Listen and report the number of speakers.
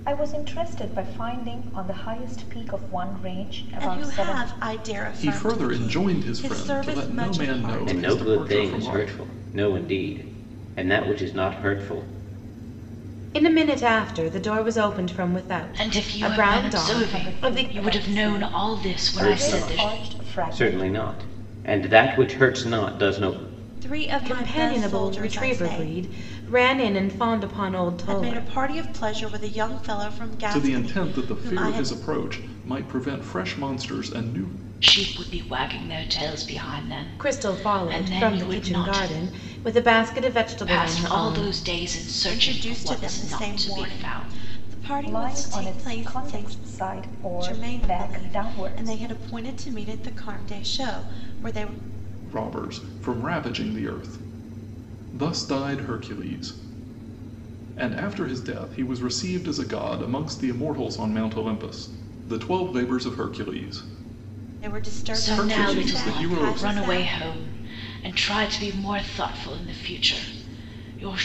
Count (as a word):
six